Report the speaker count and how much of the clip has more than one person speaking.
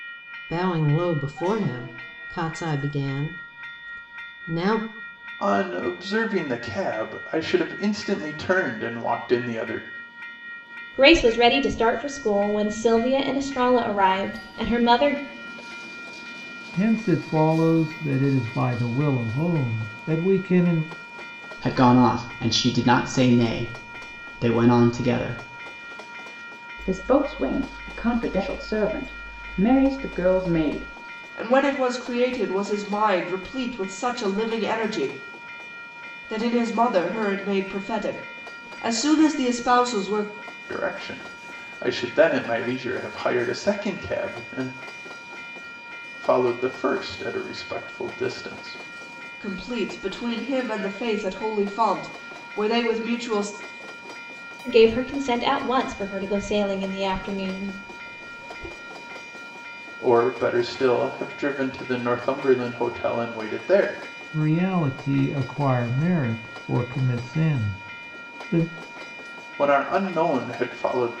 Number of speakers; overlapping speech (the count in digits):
7, no overlap